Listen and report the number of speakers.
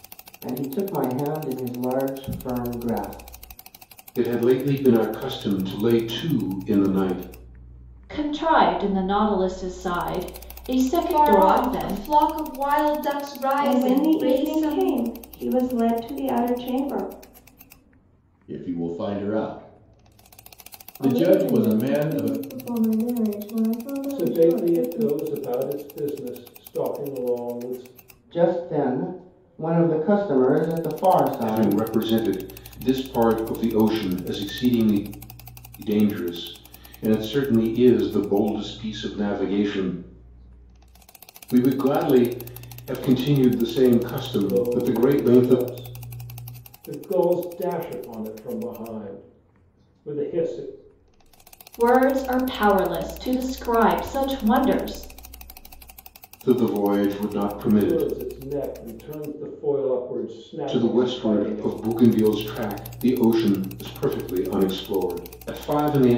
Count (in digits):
8